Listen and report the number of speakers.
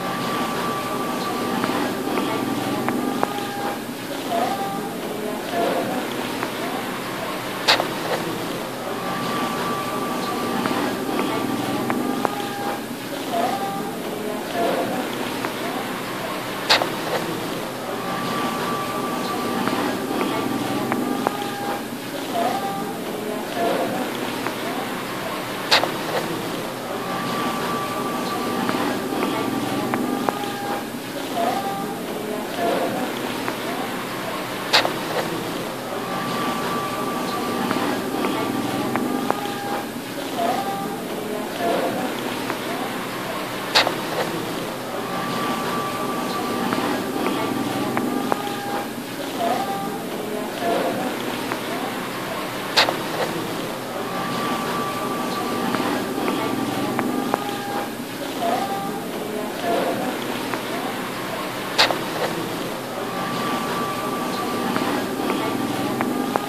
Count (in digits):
0